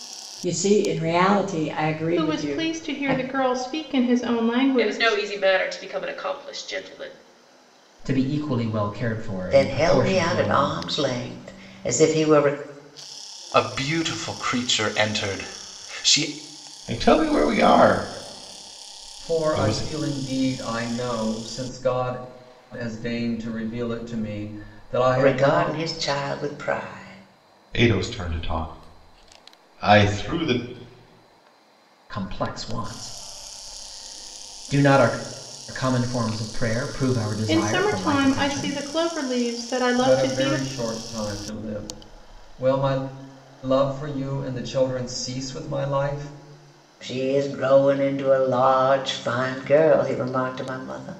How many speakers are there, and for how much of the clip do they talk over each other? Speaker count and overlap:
8, about 12%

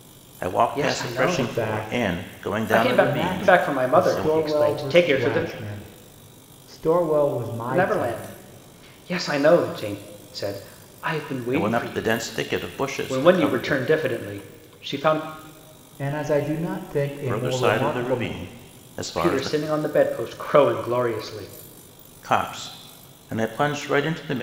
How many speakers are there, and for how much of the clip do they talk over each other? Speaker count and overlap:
3, about 35%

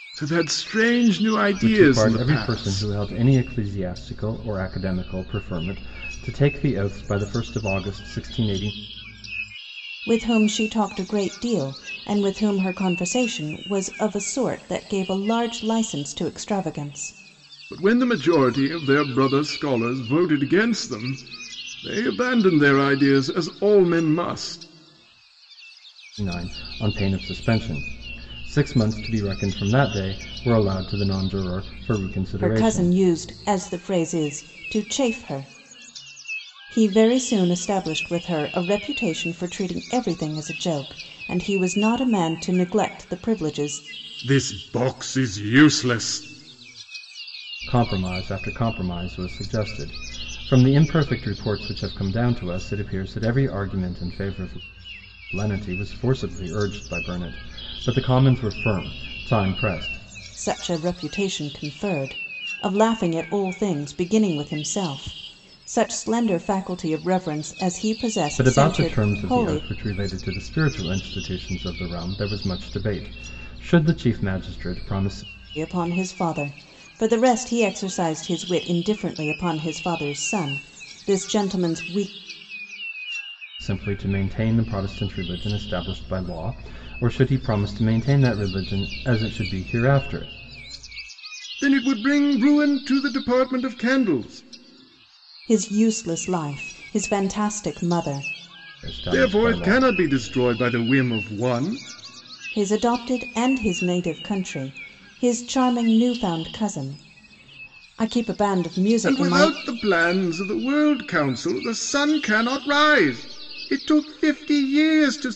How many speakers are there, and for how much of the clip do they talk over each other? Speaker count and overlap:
3, about 4%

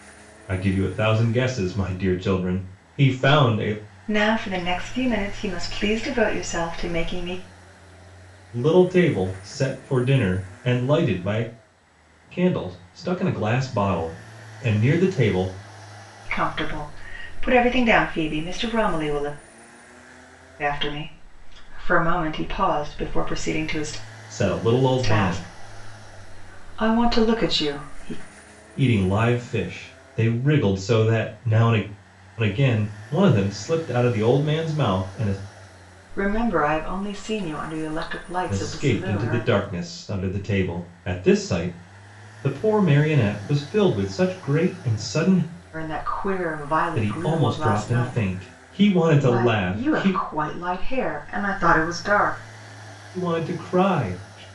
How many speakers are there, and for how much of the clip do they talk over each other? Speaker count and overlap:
2, about 7%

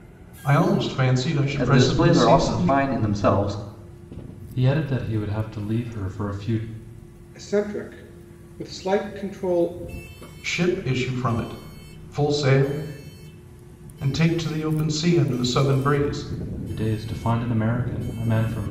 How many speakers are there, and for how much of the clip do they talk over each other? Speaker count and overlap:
4, about 6%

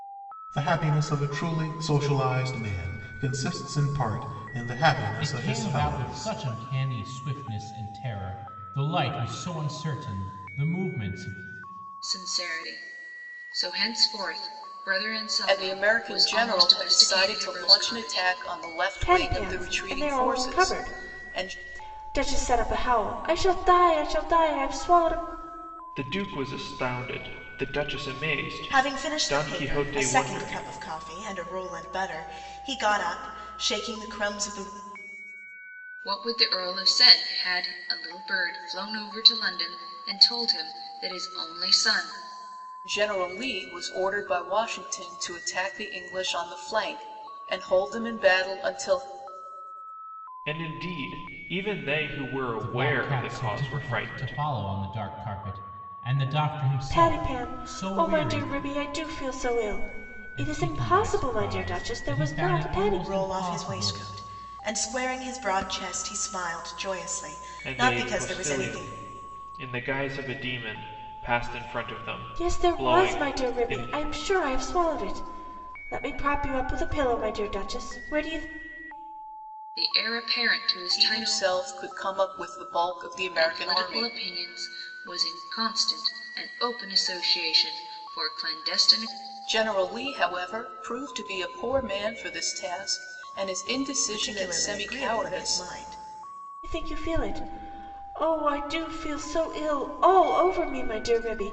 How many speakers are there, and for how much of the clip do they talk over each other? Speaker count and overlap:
7, about 22%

